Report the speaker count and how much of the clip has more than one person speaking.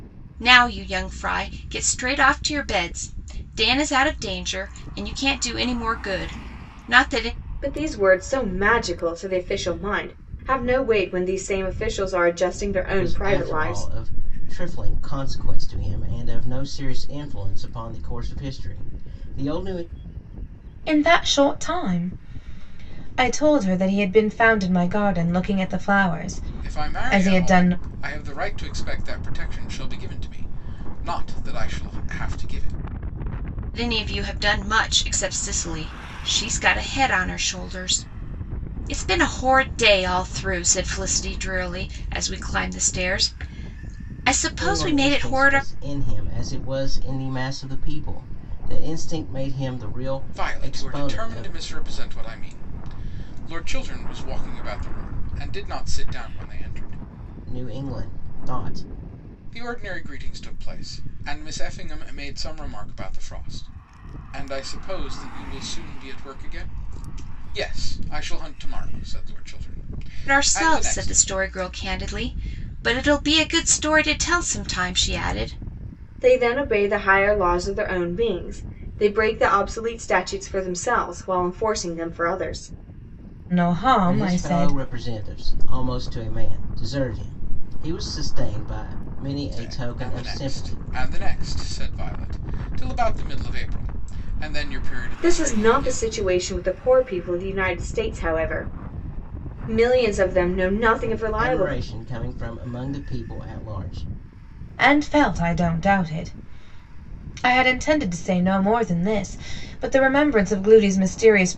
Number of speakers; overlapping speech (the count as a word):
five, about 8%